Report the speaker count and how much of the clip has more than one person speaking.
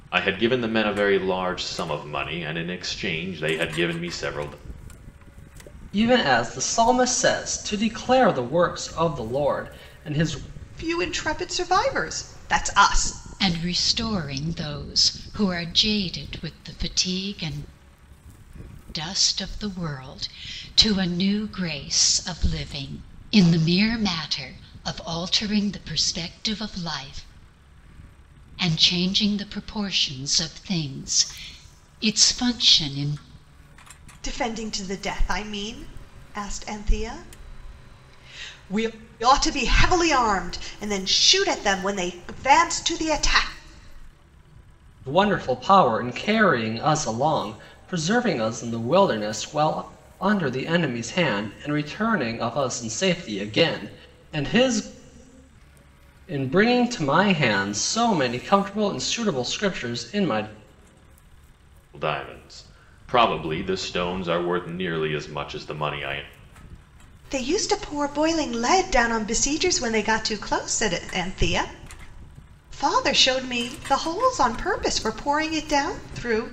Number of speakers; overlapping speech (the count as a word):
four, no overlap